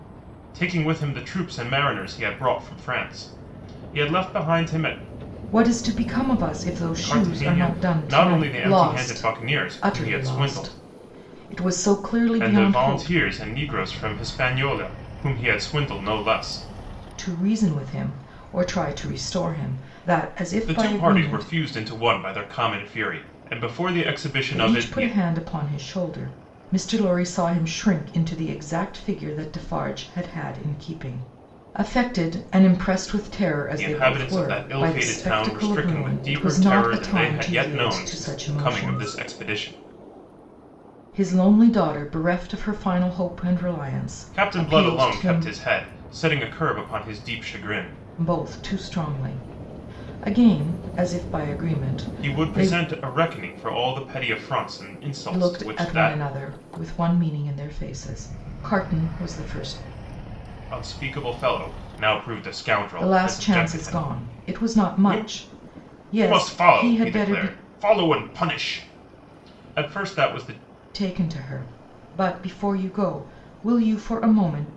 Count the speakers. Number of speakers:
2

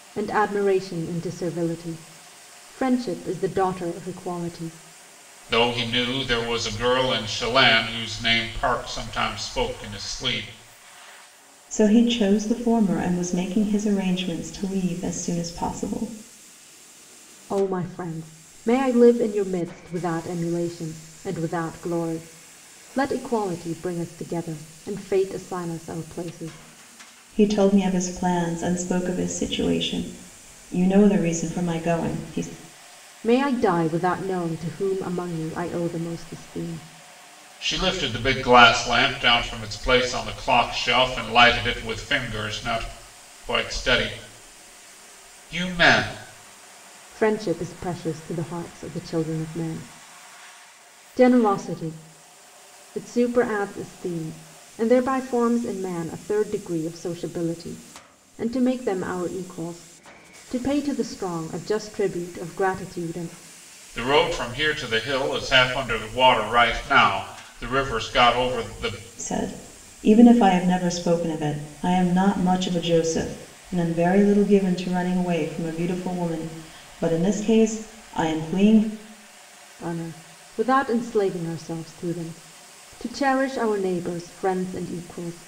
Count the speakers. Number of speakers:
3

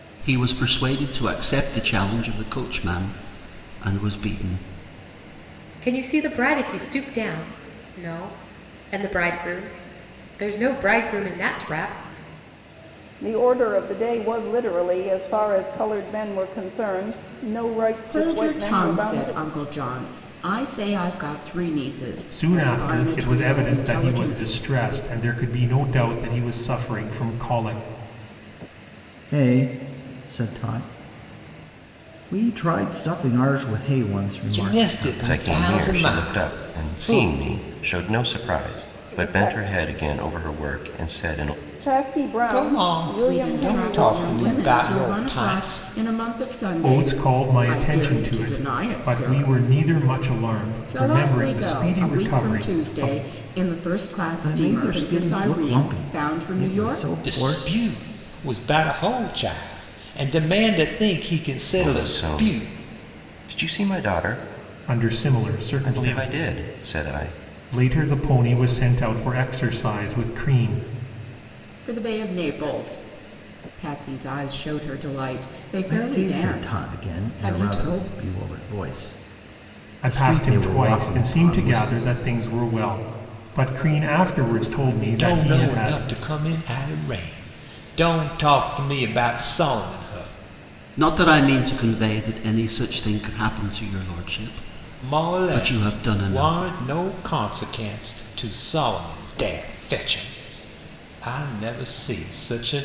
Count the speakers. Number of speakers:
8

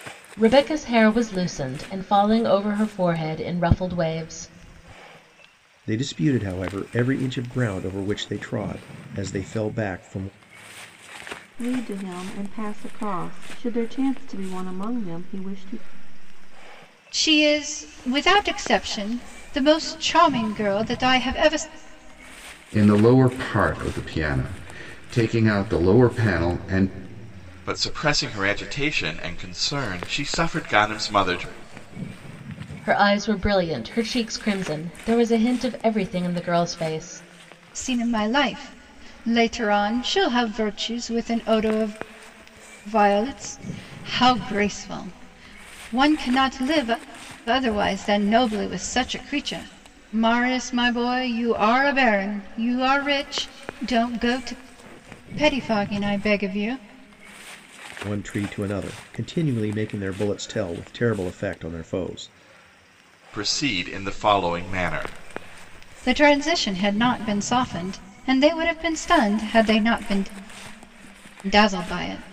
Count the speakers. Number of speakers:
6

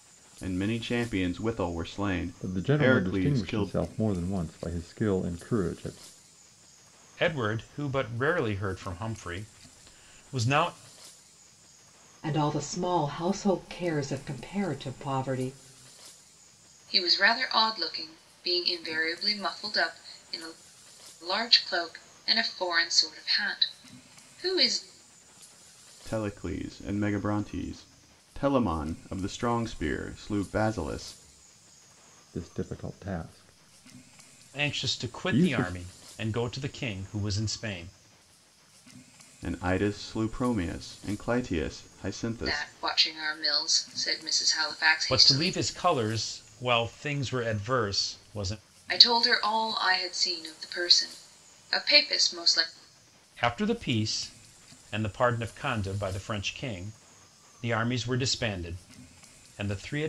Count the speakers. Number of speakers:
5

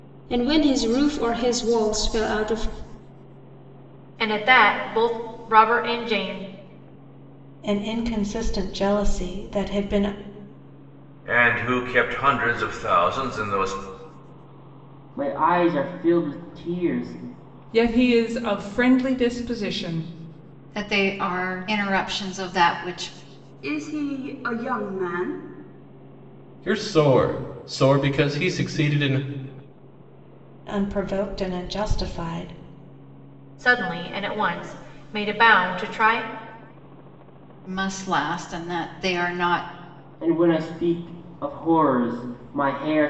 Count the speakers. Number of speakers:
9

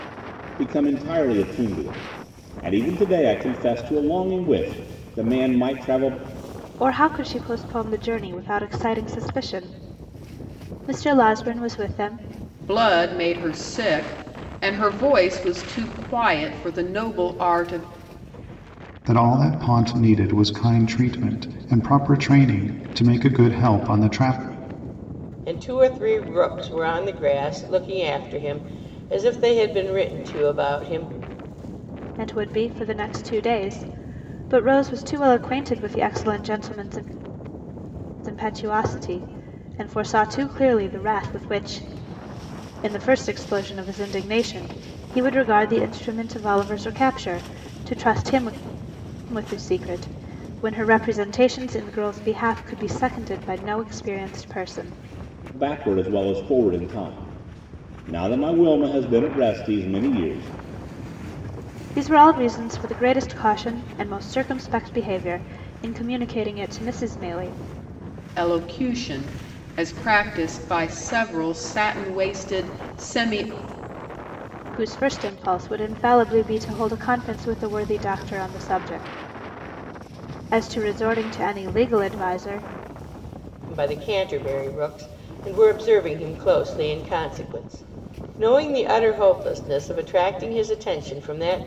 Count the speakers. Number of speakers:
5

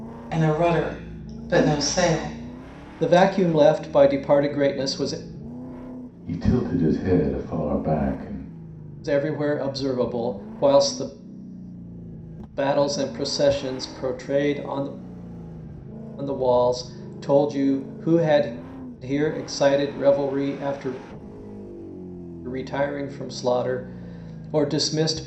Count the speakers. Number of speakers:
3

